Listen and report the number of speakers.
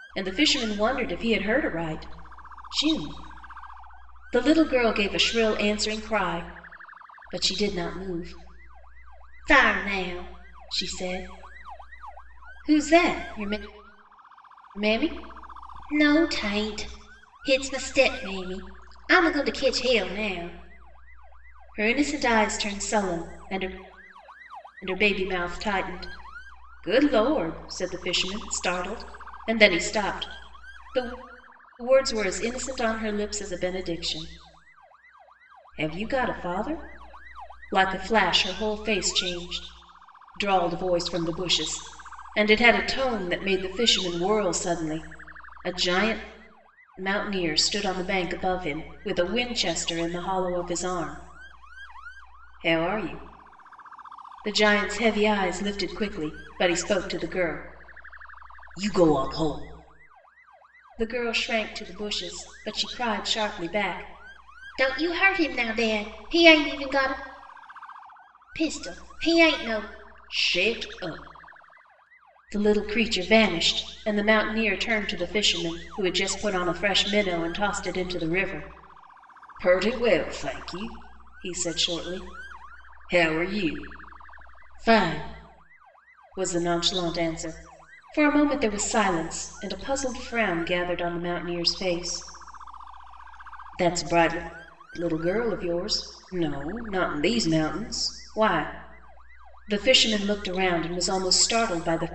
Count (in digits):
1